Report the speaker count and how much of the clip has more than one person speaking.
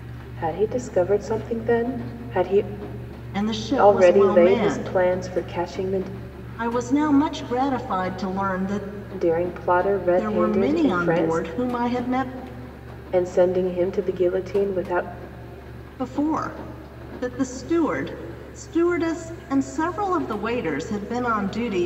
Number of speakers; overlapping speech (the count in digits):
2, about 12%